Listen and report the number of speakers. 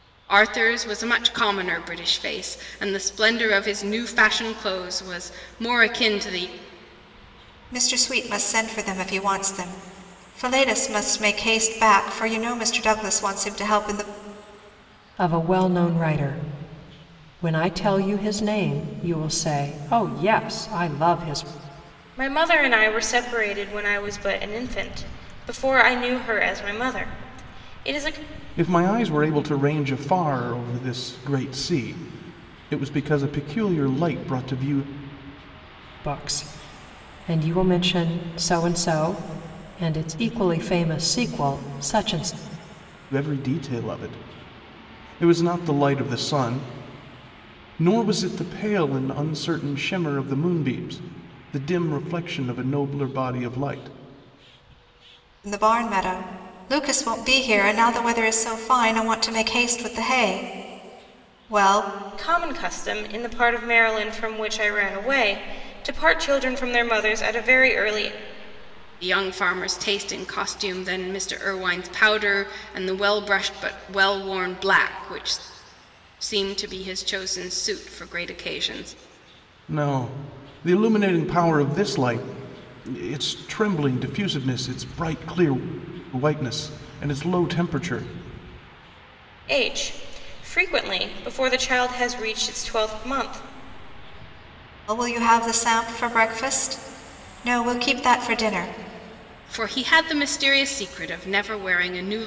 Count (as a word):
five